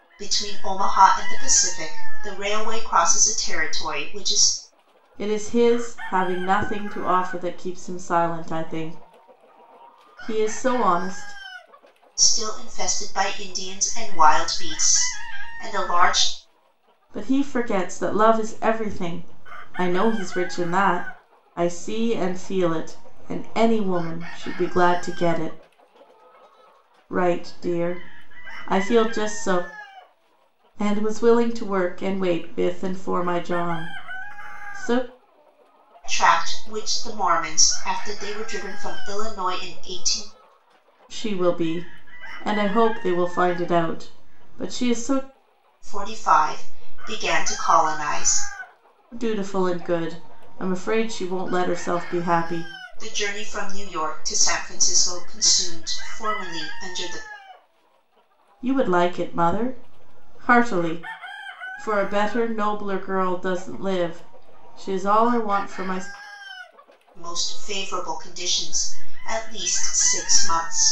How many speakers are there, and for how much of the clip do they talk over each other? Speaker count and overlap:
2, no overlap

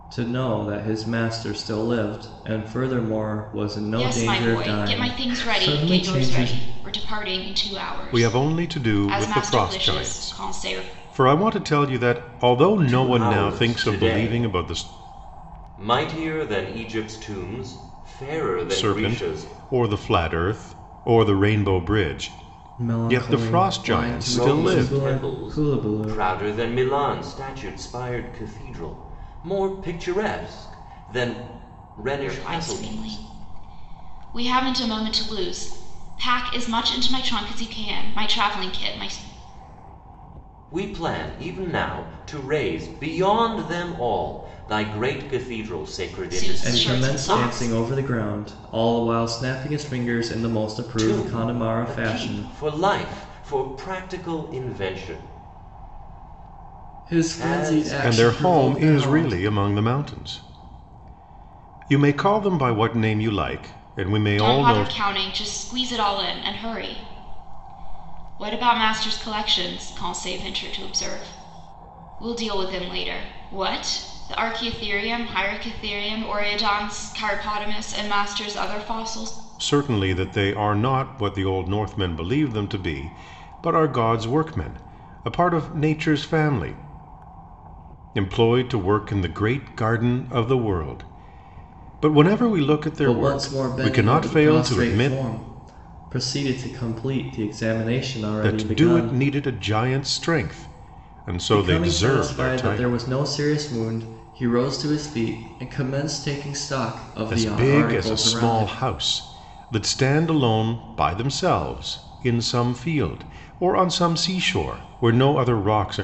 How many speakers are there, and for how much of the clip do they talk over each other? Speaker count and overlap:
4, about 21%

